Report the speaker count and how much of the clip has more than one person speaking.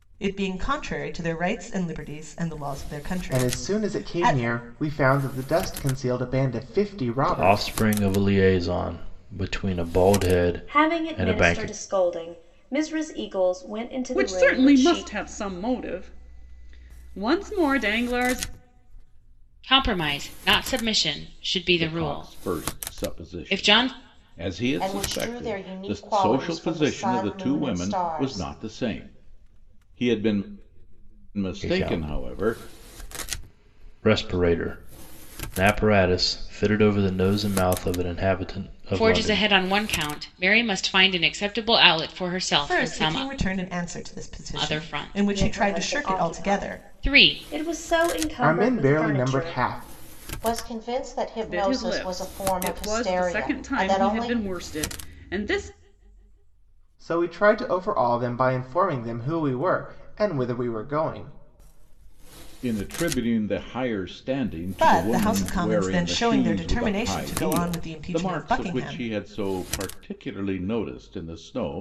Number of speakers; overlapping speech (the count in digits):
8, about 32%